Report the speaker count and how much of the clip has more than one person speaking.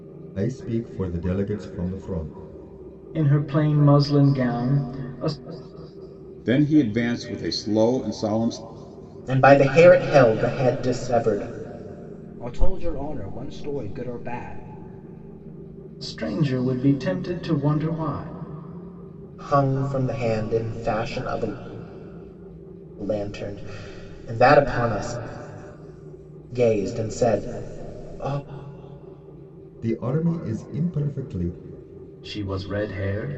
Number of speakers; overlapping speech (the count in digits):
5, no overlap